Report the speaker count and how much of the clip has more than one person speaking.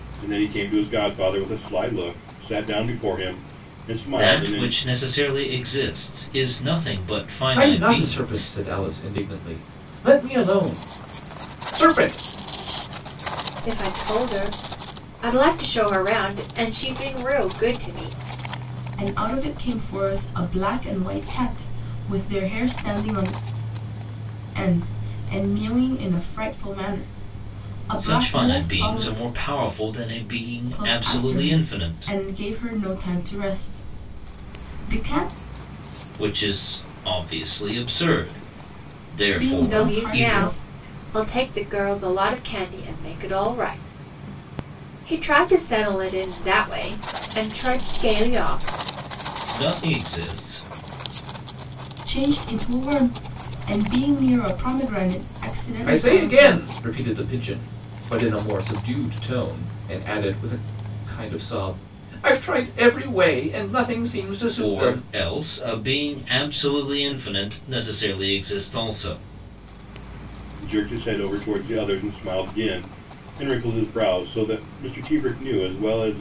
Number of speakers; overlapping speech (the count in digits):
5, about 9%